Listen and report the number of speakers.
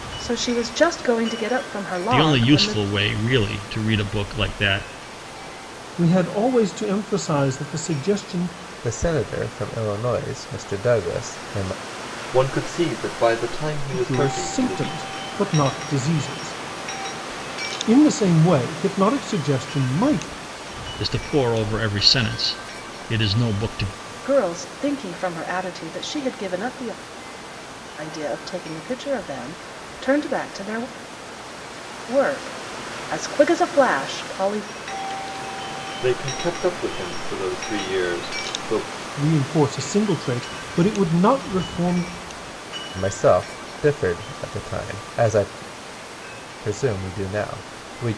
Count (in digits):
5